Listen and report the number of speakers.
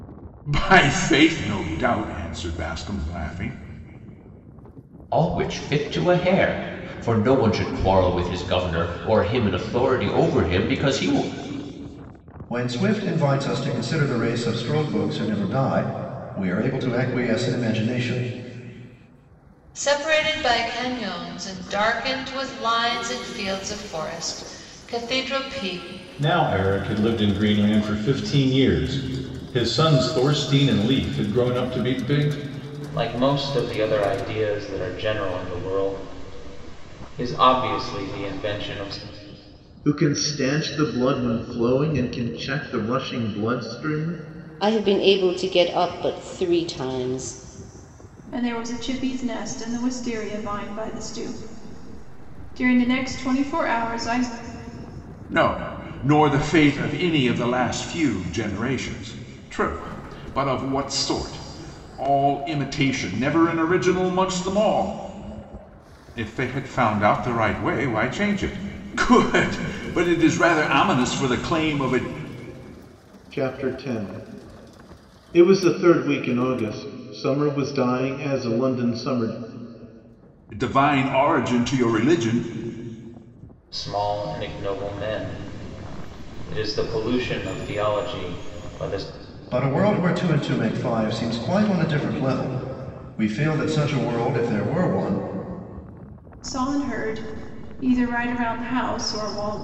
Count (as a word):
nine